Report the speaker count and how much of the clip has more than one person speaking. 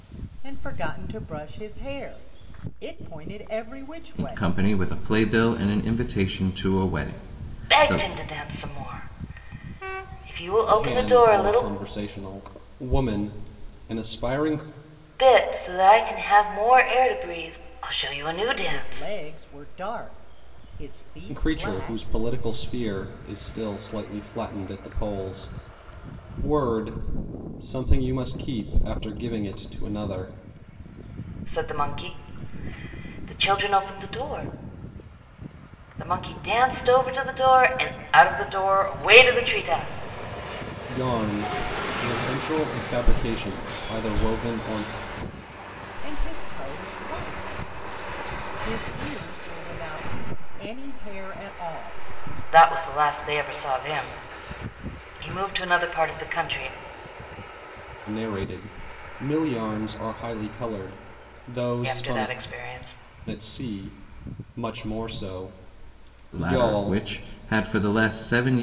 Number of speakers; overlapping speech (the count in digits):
4, about 6%